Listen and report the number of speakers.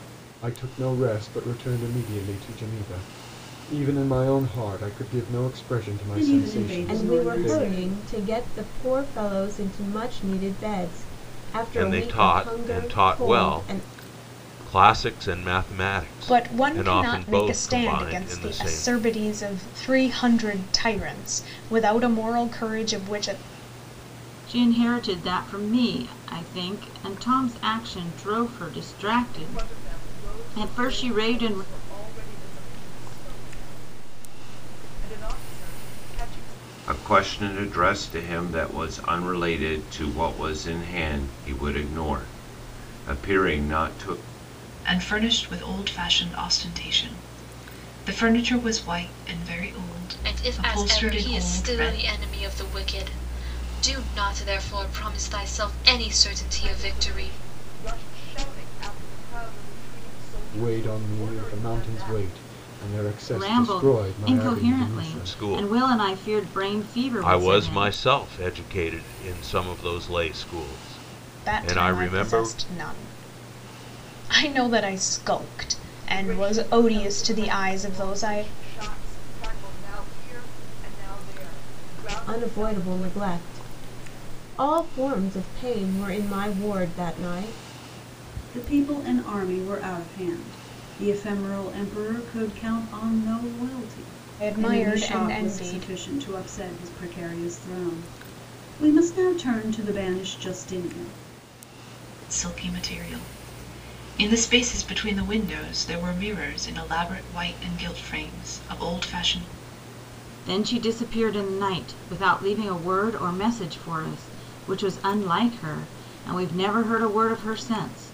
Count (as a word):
ten